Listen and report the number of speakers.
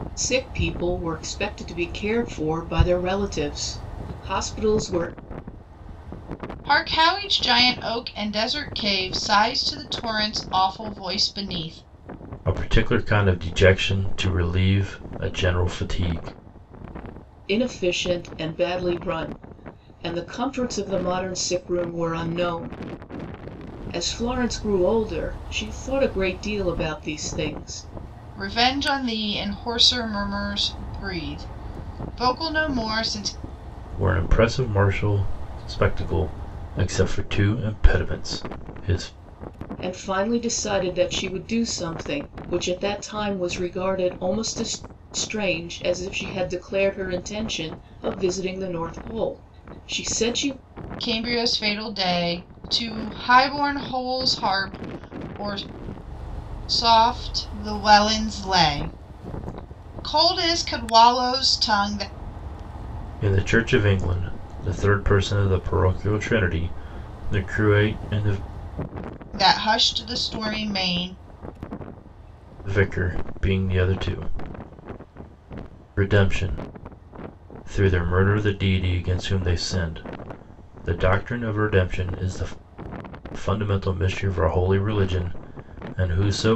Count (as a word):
three